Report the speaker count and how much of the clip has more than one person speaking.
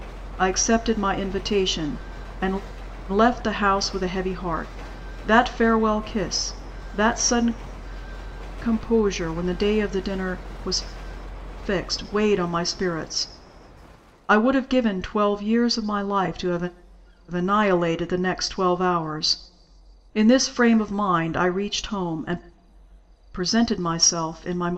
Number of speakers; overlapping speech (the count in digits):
1, no overlap